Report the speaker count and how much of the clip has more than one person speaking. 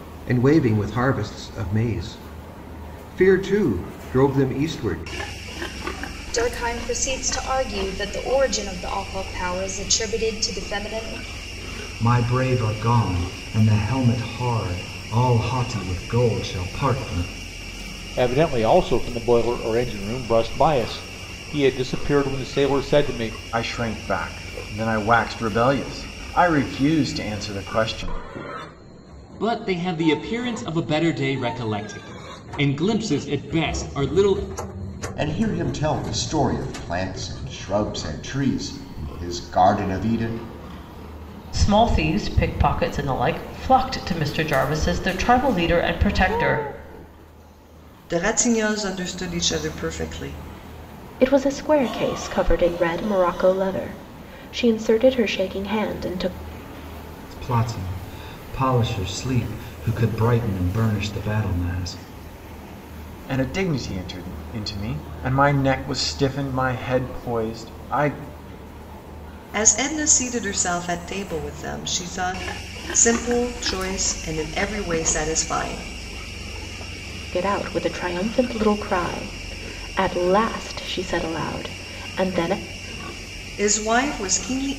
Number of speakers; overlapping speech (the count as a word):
ten, no overlap